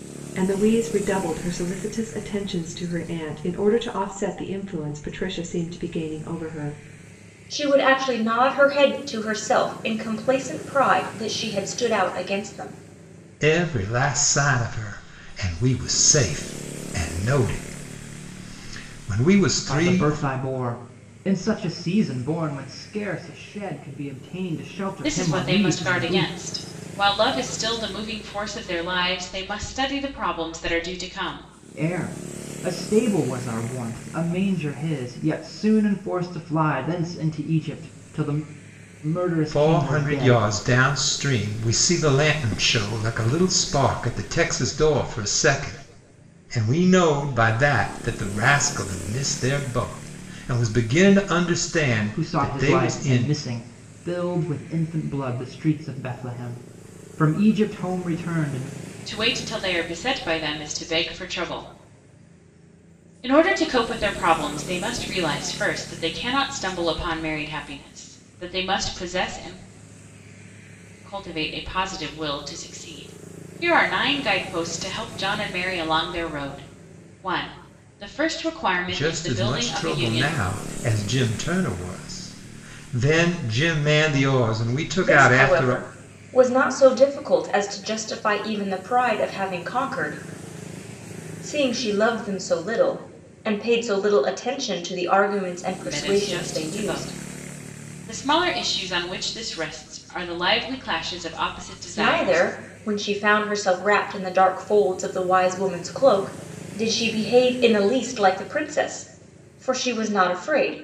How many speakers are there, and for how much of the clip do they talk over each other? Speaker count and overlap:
five, about 8%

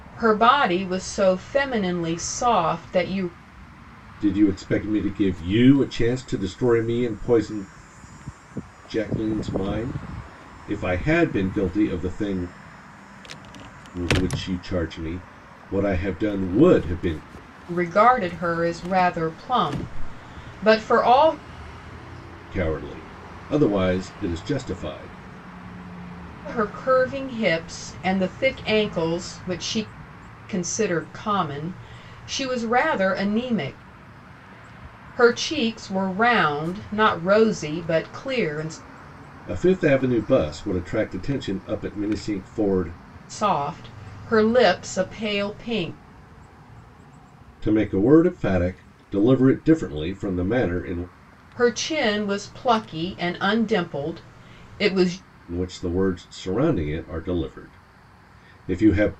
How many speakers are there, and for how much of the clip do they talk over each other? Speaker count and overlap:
two, no overlap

